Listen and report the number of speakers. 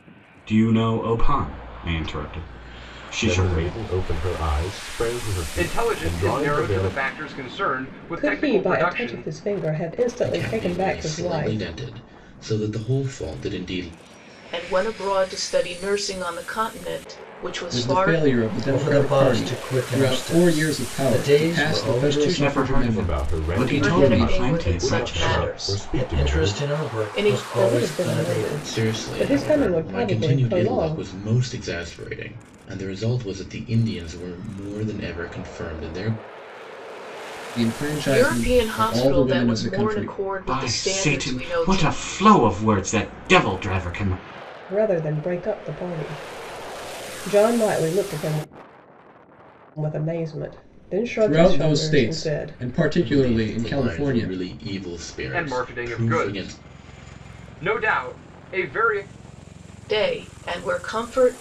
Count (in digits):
8